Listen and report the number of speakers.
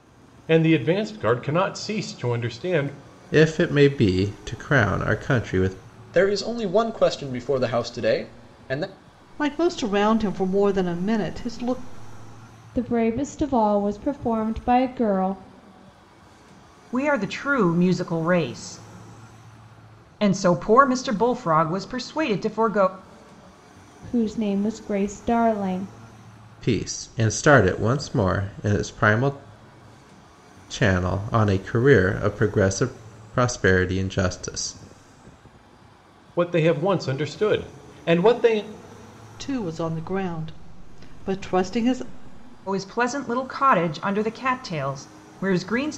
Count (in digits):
6